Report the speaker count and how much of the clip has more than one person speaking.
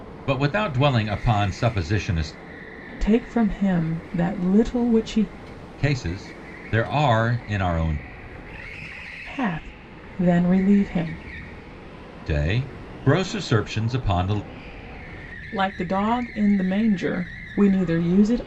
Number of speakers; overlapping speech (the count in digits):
2, no overlap